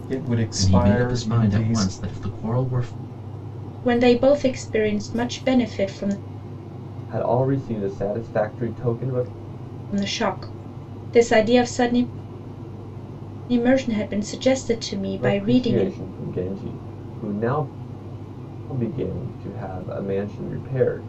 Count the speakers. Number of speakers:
four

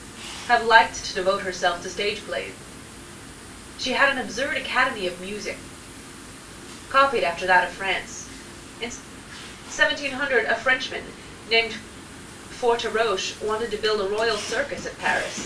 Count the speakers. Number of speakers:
one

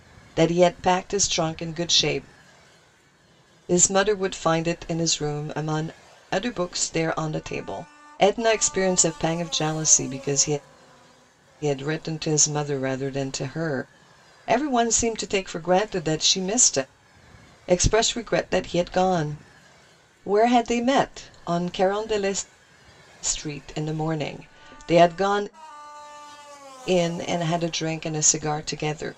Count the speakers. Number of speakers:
one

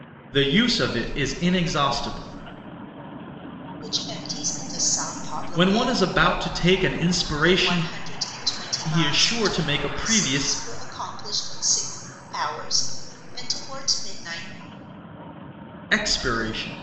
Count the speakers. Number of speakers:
two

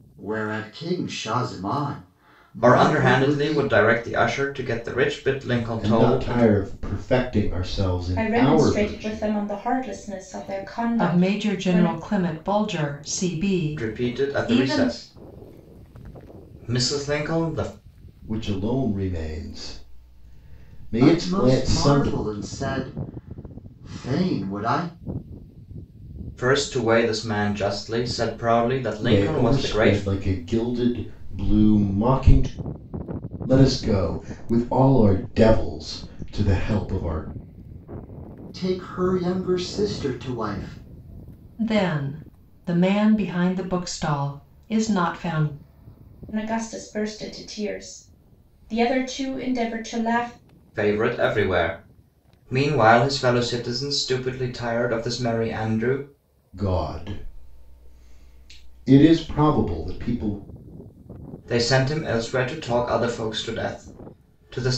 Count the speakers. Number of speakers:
five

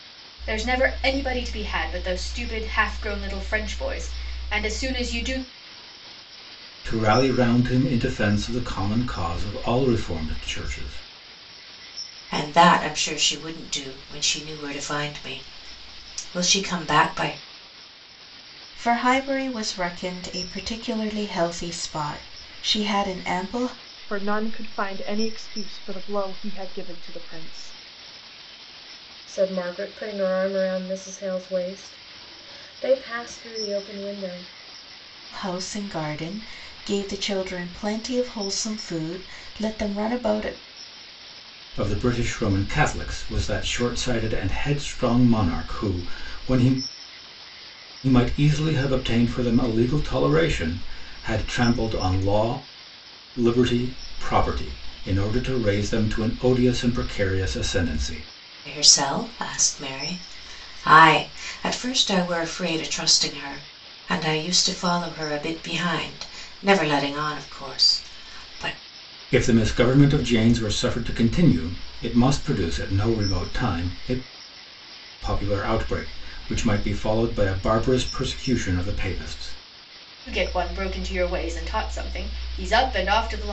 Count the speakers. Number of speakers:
six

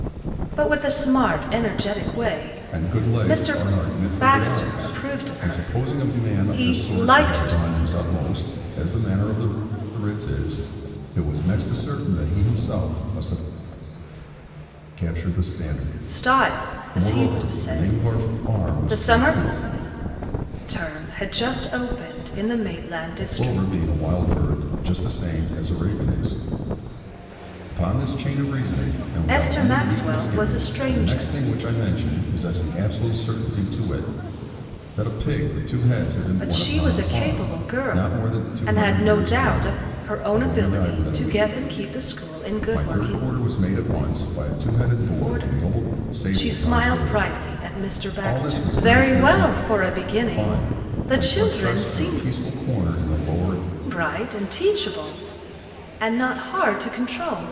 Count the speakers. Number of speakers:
two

